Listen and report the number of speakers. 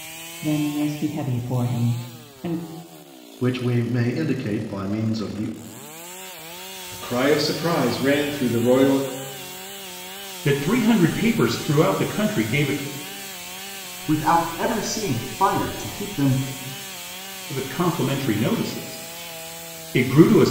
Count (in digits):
5